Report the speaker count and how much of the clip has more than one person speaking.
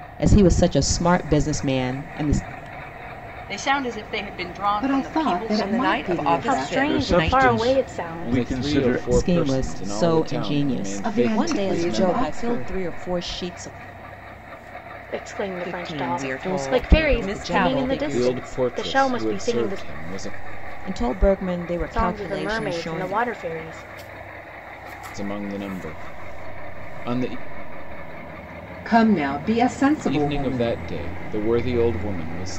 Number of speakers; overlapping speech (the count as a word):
seven, about 44%